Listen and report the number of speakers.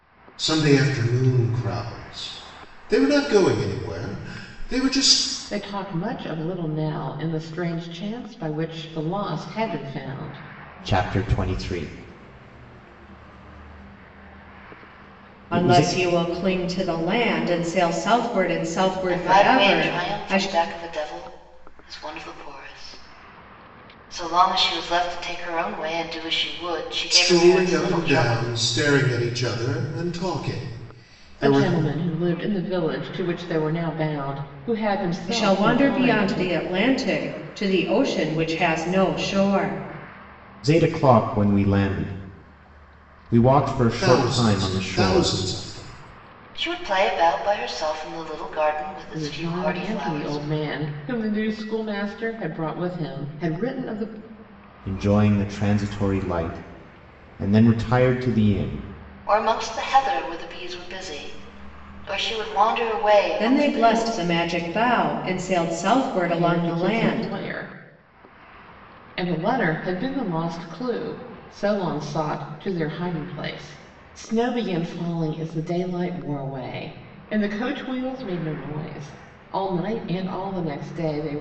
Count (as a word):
five